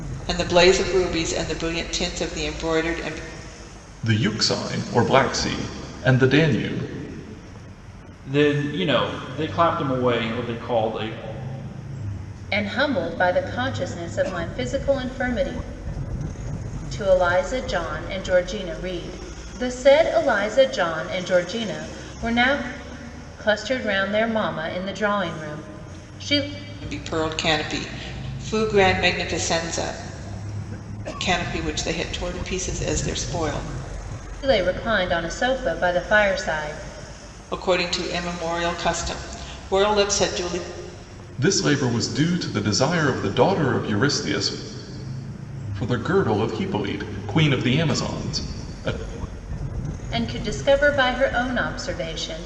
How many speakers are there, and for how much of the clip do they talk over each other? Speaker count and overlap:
4, no overlap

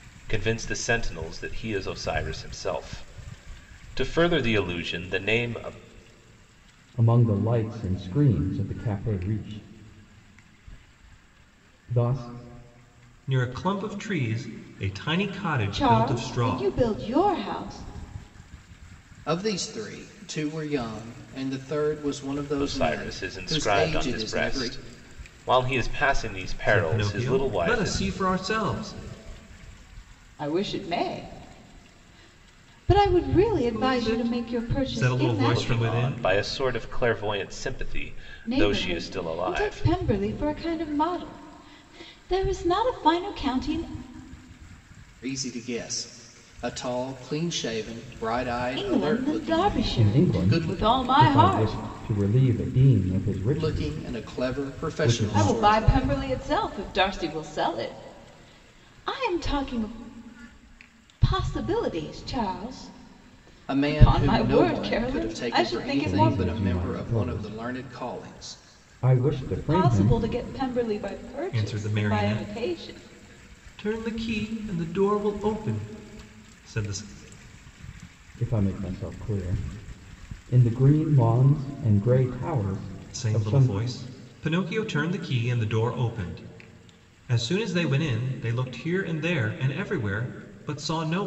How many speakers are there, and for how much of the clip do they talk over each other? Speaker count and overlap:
5, about 24%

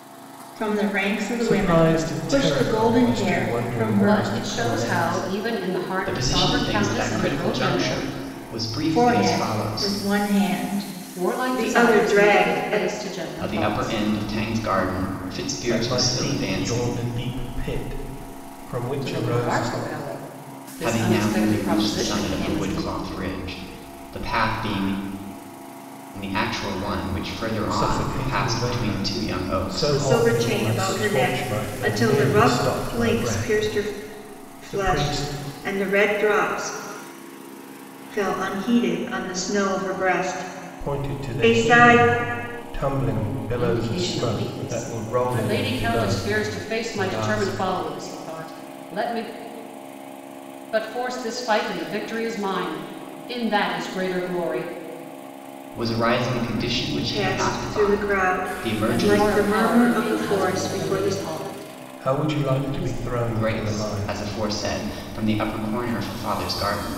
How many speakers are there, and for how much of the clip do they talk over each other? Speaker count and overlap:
4, about 48%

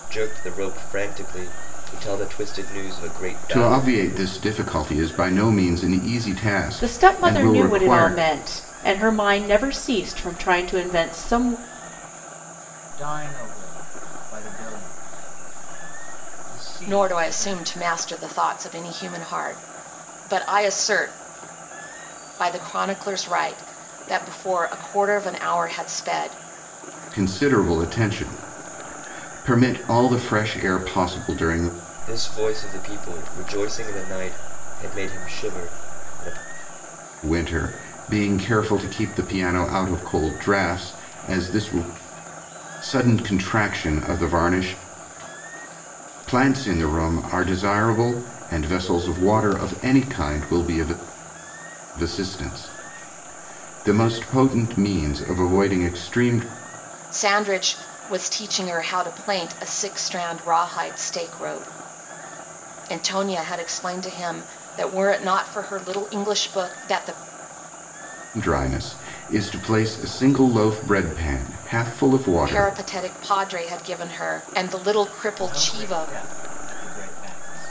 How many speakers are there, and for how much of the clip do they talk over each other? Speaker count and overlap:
5, about 5%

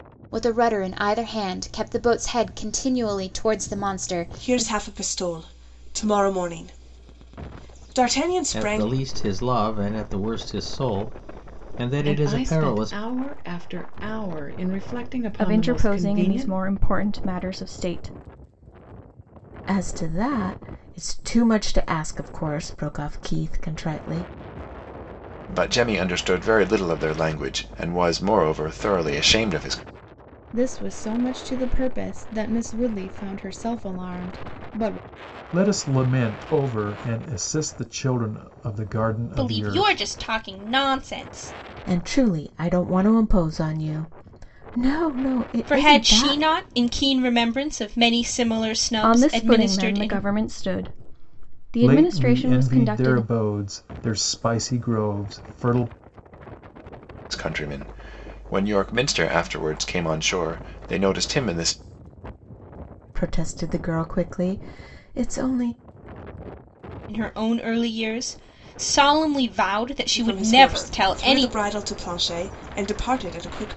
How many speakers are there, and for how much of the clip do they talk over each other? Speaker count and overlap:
10, about 12%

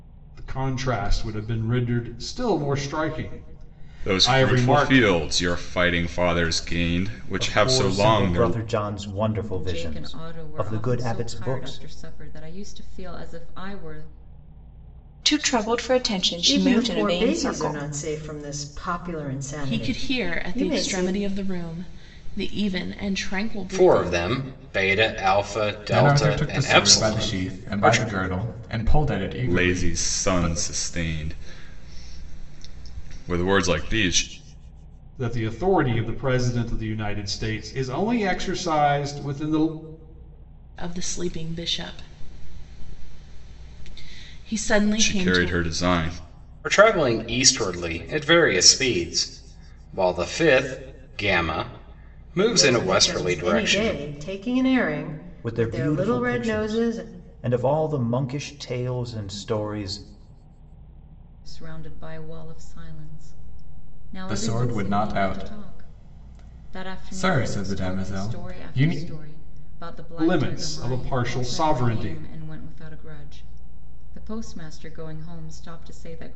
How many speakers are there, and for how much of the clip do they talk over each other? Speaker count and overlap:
9, about 28%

